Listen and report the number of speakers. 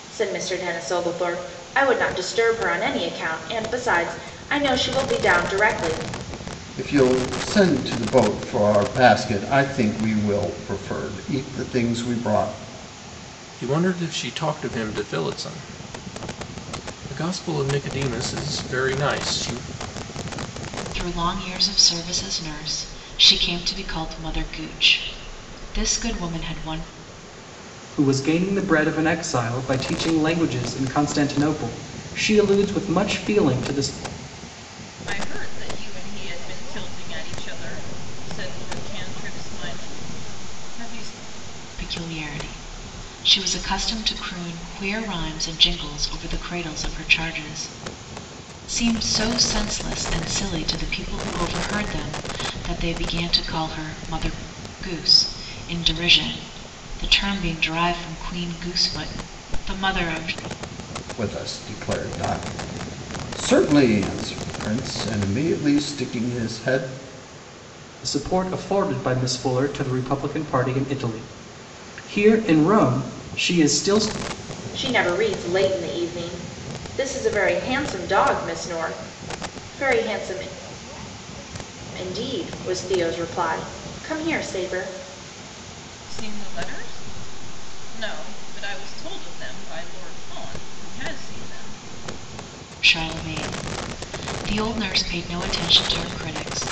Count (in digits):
6